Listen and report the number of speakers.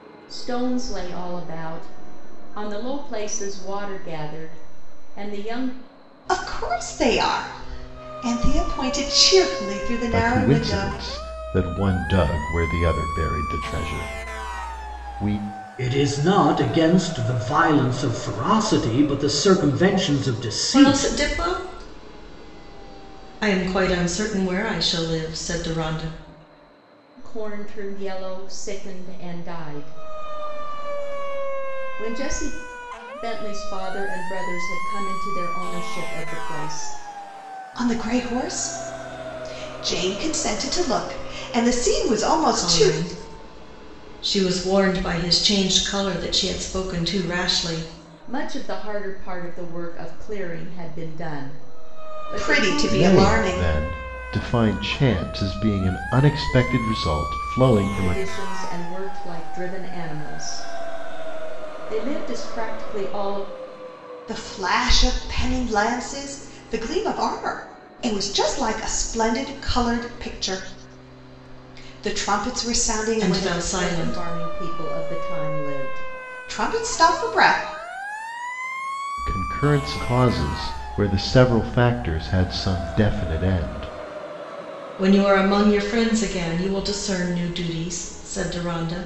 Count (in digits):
5